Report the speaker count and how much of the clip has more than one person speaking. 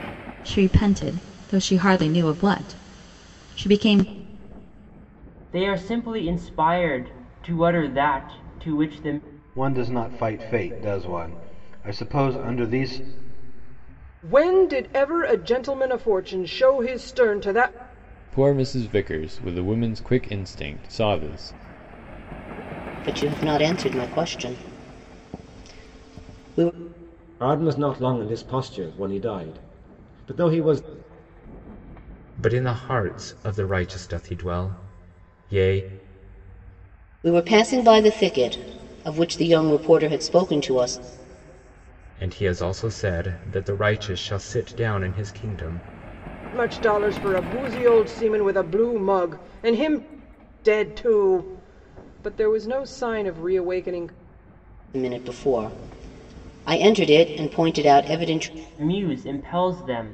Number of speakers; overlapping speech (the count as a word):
eight, no overlap